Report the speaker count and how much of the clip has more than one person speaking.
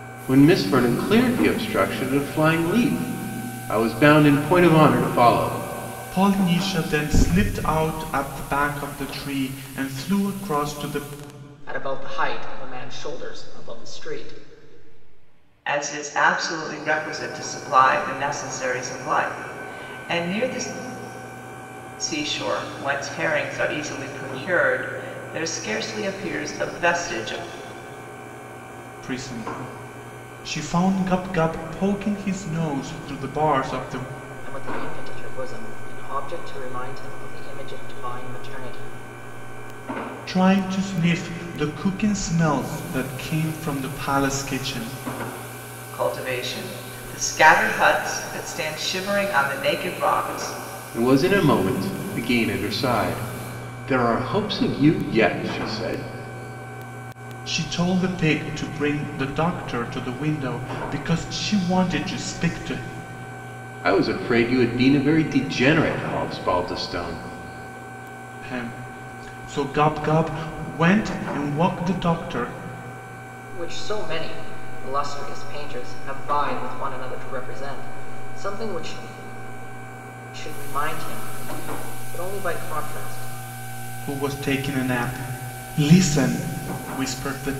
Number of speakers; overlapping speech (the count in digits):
4, no overlap